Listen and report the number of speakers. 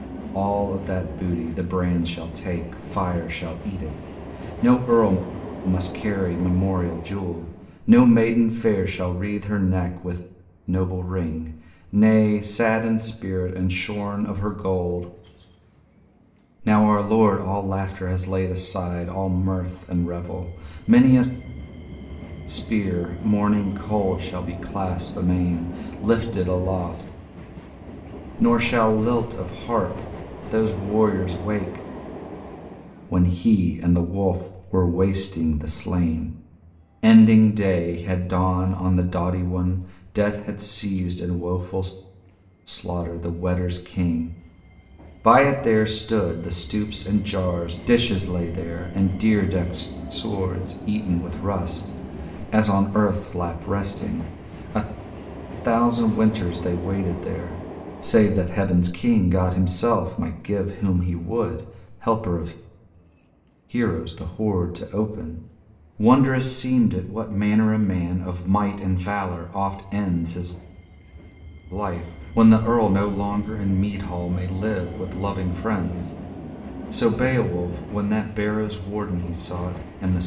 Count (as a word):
one